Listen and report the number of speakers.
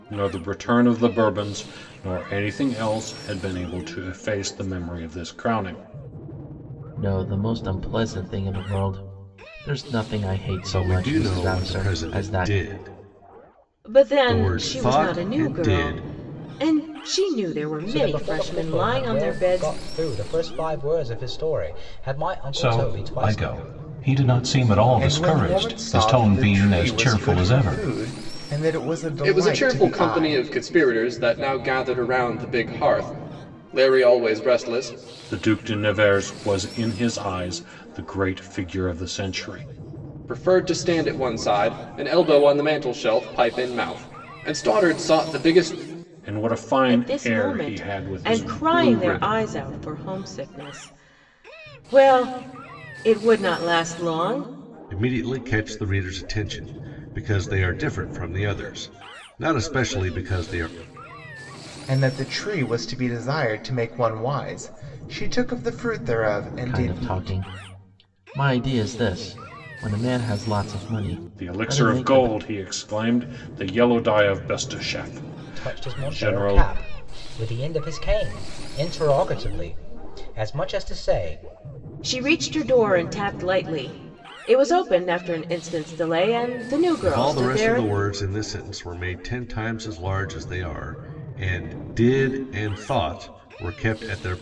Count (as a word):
eight